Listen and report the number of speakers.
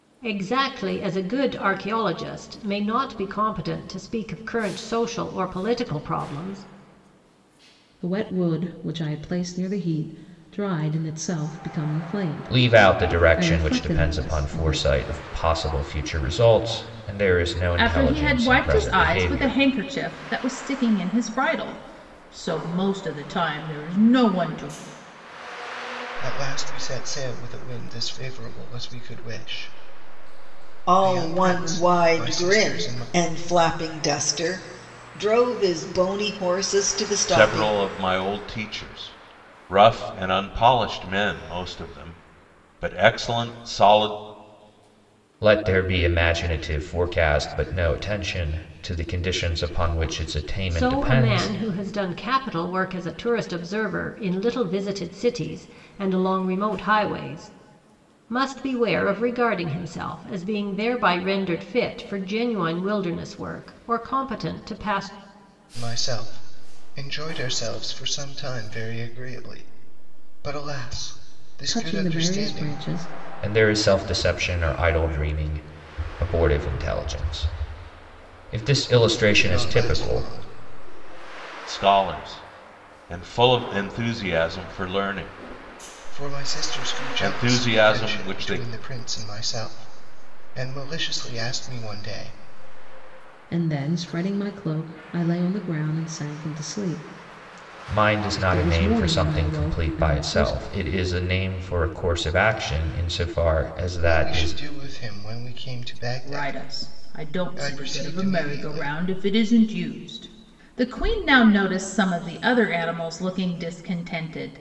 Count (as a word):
seven